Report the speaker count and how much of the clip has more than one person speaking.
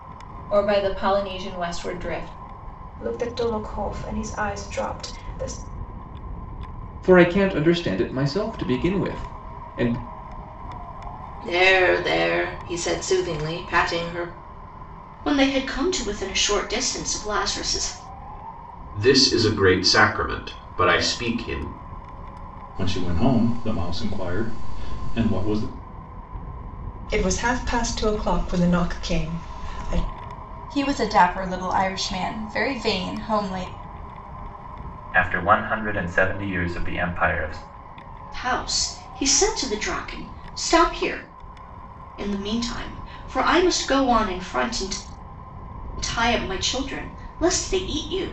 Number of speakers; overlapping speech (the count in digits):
10, no overlap